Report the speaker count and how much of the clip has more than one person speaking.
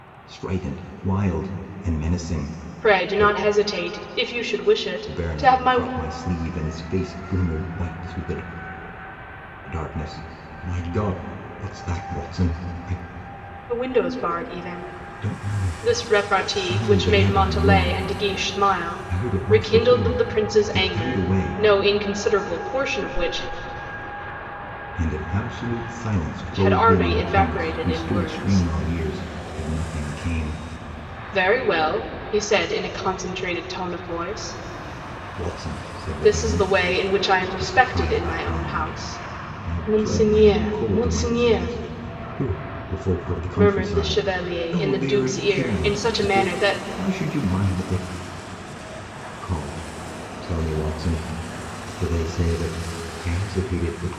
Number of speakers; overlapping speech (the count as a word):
two, about 31%